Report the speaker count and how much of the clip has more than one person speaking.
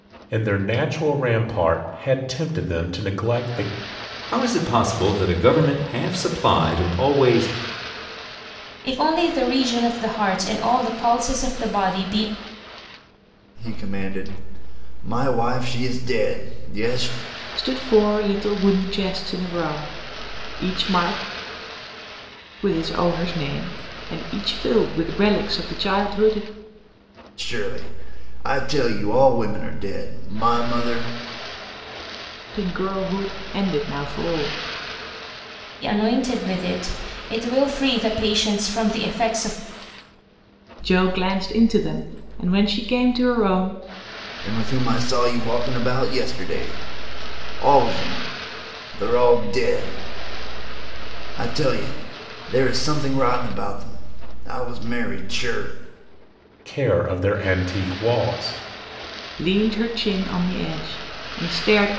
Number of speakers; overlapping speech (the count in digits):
5, no overlap